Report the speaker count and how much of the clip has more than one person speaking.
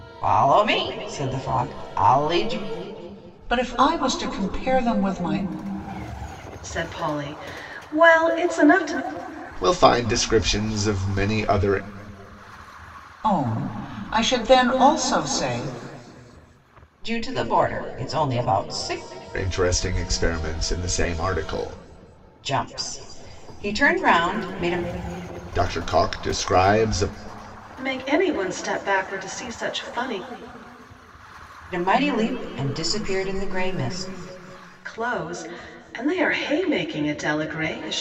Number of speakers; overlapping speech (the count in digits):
4, no overlap